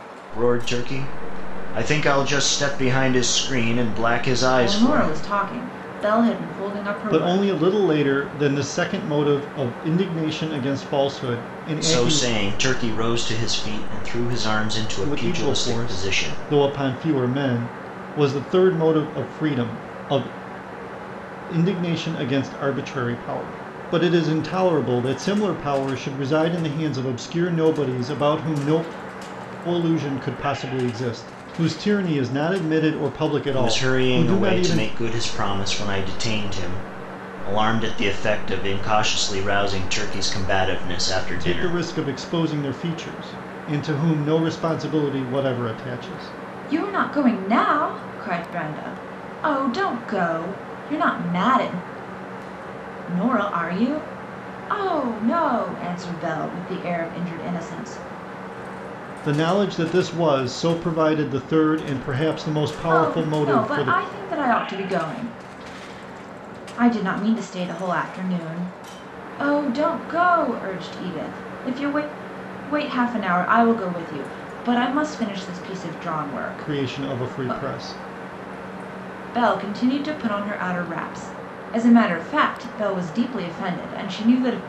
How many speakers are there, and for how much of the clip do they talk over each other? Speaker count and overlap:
3, about 8%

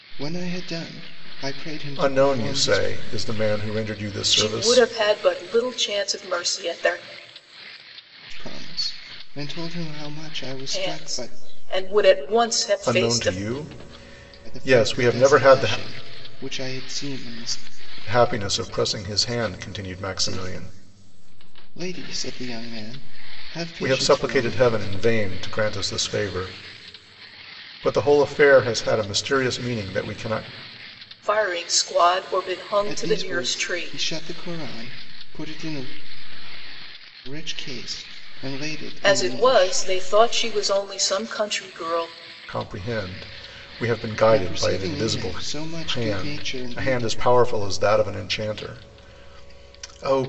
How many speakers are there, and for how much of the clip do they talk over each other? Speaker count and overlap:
3, about 20%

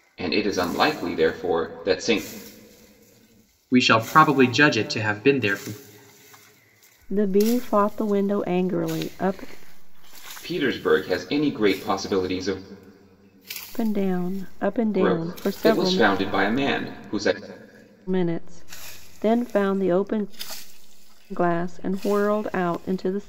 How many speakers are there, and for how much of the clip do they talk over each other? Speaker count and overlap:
3, about 5%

